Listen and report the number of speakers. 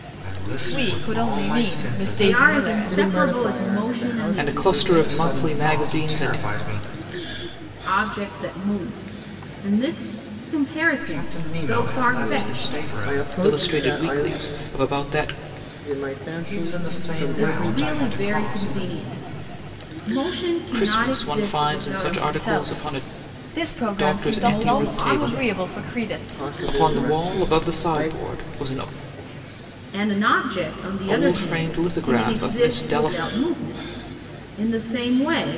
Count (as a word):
five